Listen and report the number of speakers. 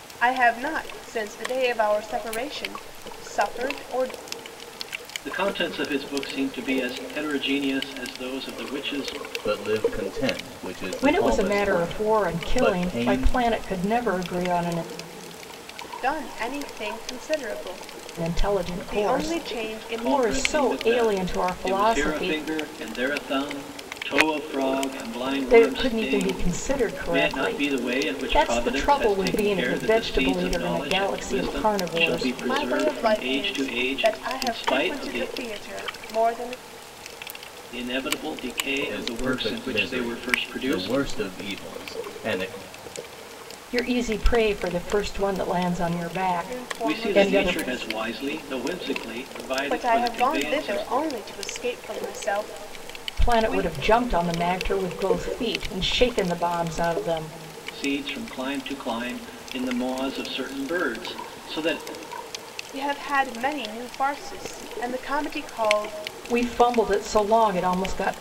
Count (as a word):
four